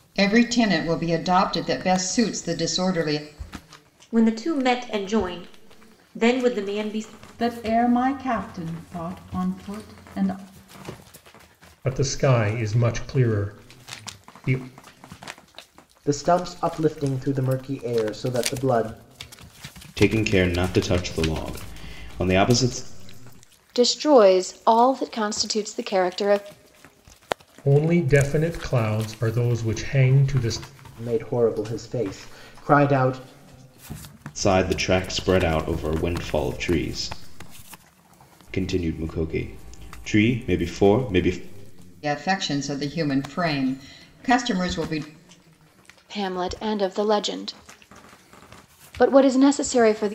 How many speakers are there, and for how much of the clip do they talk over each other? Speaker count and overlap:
seven, no overlap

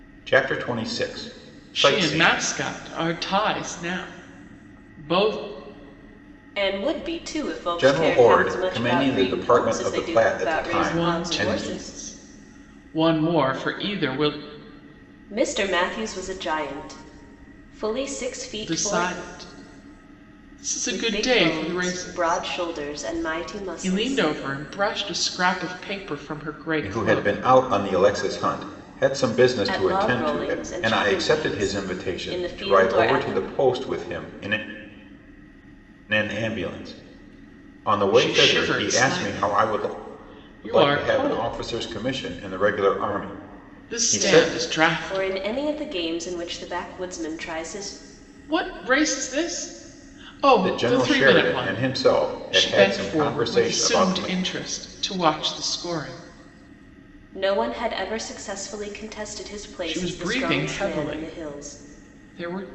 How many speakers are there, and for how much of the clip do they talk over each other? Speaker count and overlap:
three, about 33%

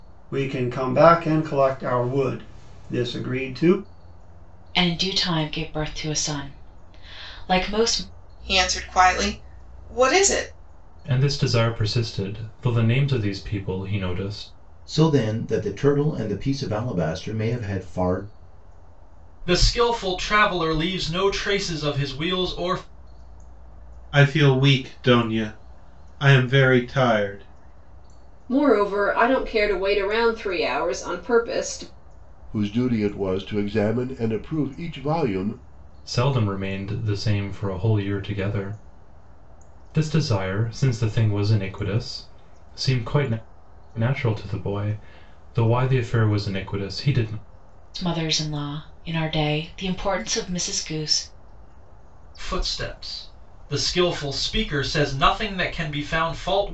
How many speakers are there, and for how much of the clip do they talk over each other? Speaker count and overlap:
nine, no overlap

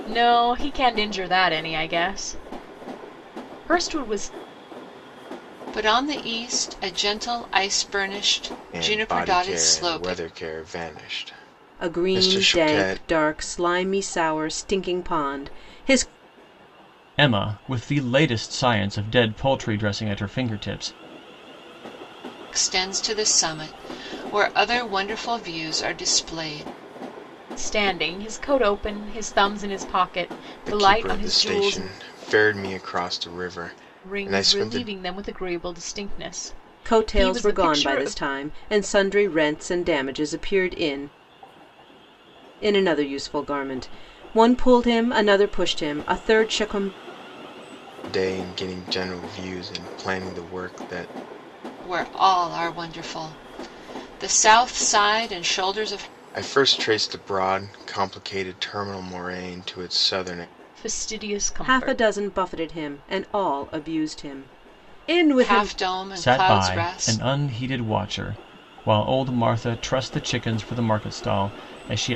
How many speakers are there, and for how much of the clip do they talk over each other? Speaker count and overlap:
five, about 12%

